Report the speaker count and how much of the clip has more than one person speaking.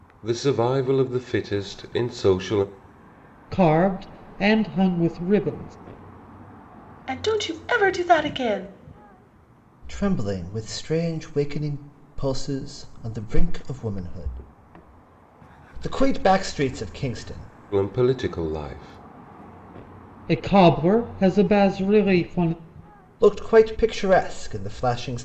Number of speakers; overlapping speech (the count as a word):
four, no overlap